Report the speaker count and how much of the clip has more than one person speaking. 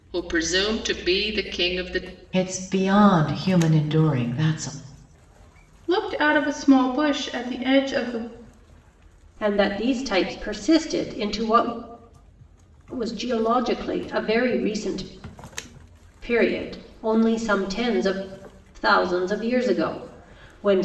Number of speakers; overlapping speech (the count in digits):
4, no overlap